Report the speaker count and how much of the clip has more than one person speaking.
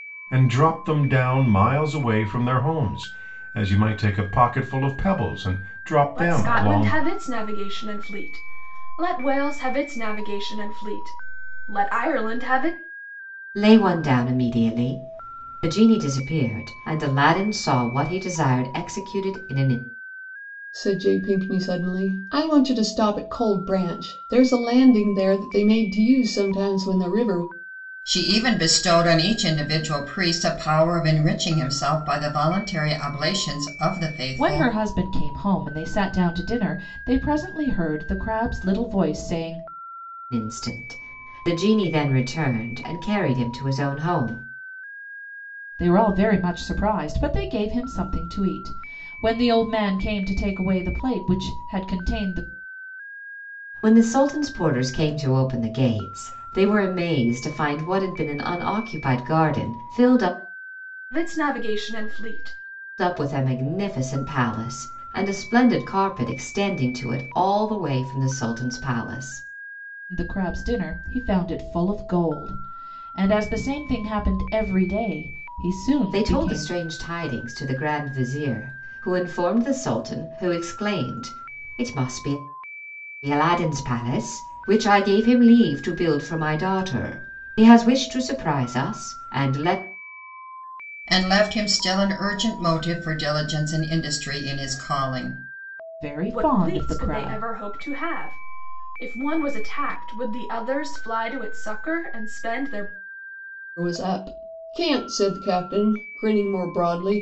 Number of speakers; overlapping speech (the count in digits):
6, about 3%